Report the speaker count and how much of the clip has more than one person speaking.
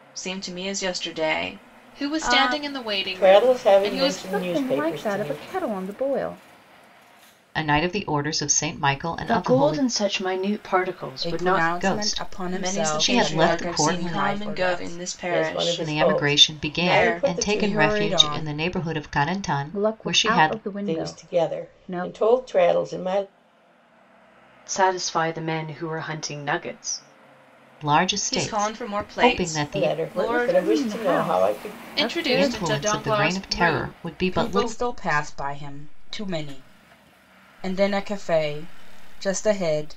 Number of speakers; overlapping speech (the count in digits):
7, about 48%